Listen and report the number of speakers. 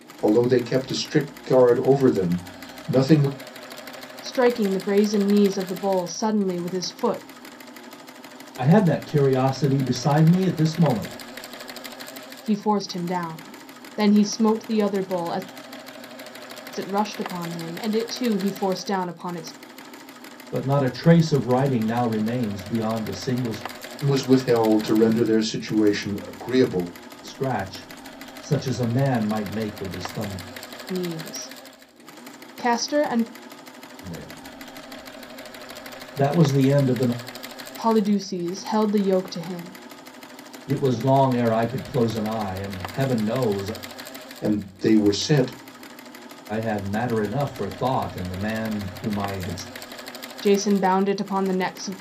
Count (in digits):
3